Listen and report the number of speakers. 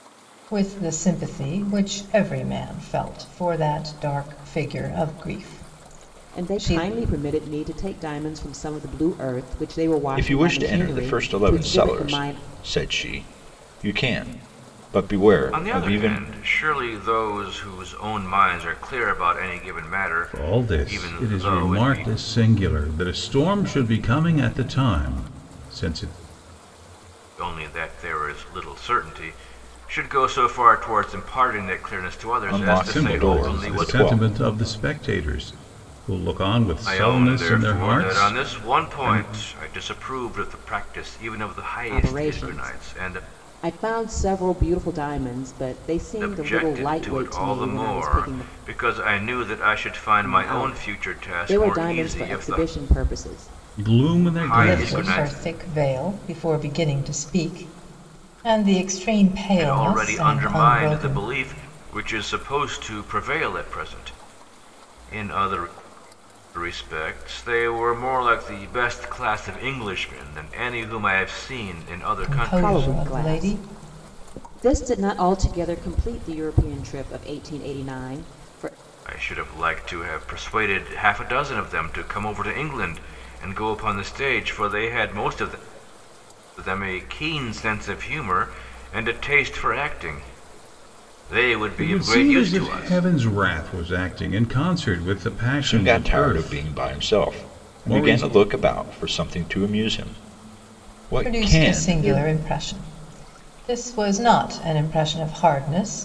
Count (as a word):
five